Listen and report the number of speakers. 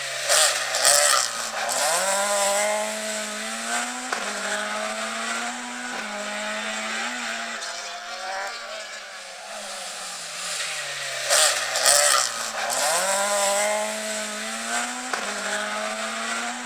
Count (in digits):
0